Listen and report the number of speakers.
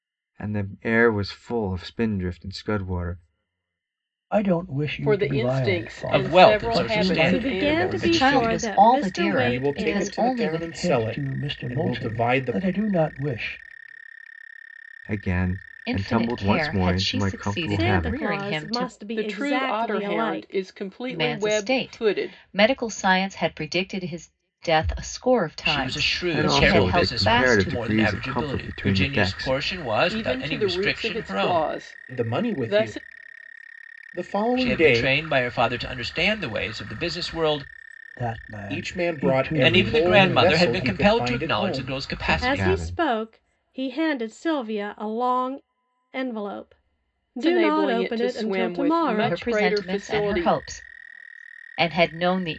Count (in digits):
7